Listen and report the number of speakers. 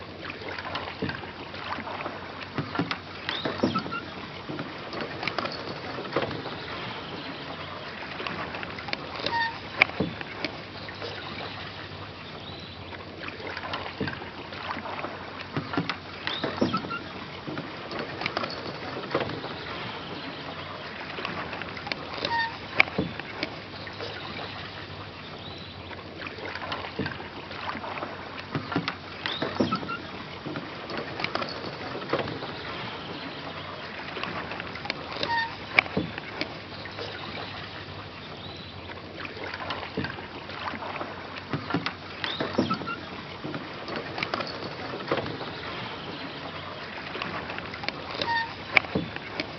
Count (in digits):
0